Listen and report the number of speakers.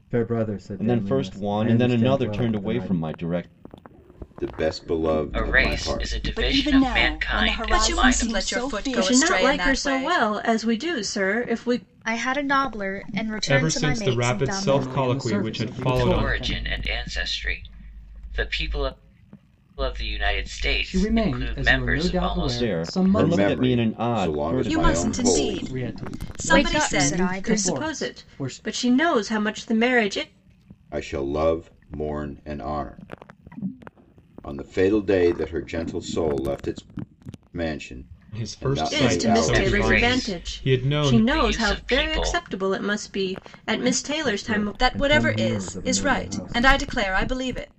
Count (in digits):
10